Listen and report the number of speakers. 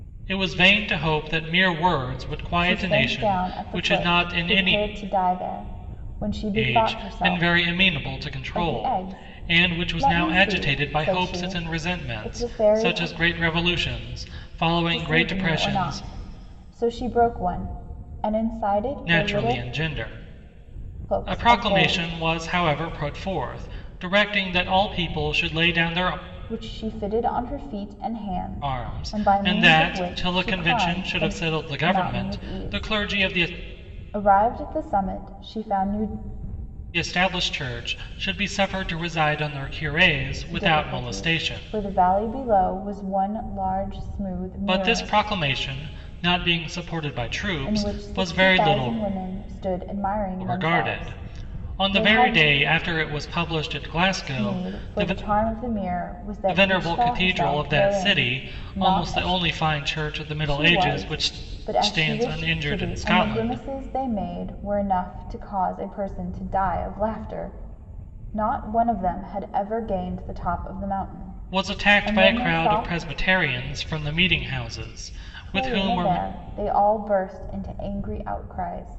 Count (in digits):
2